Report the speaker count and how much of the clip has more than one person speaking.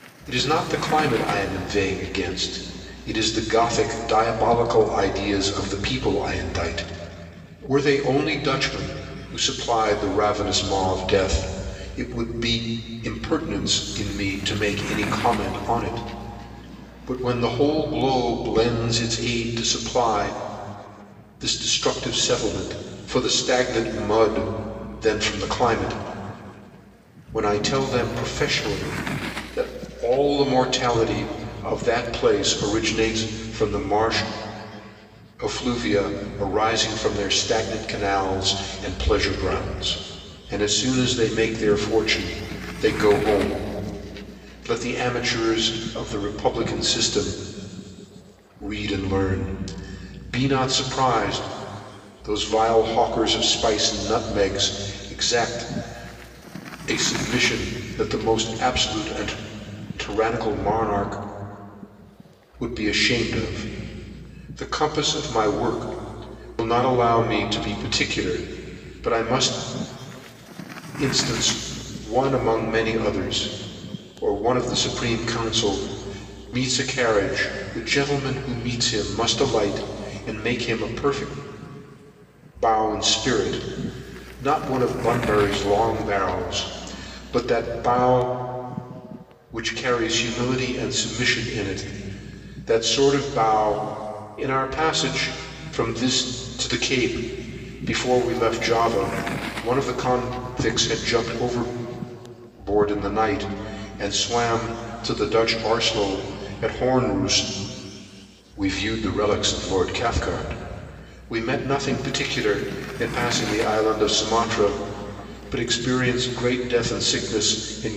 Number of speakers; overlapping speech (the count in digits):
1, no overlap